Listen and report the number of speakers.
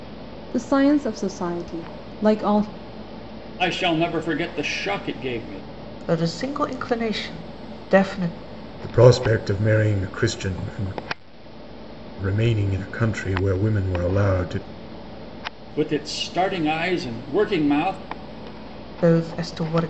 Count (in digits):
4